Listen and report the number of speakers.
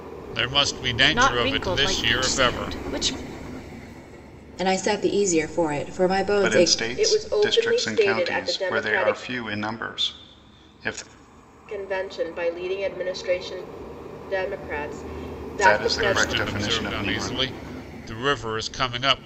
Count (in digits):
5